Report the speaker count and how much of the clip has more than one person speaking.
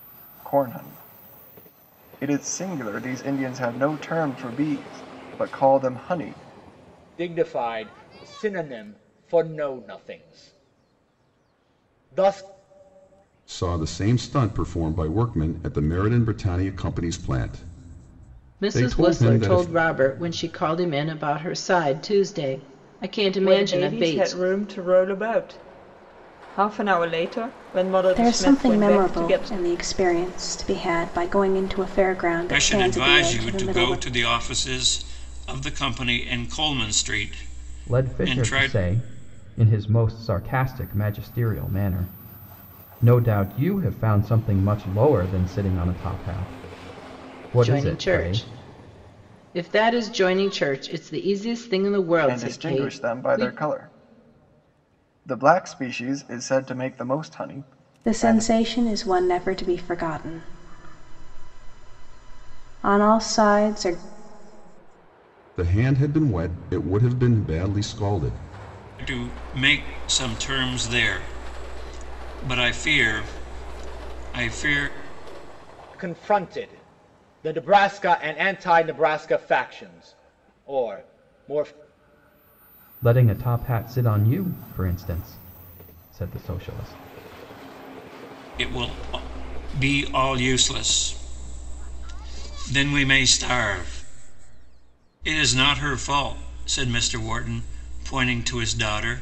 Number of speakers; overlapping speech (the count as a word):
eight, about 9%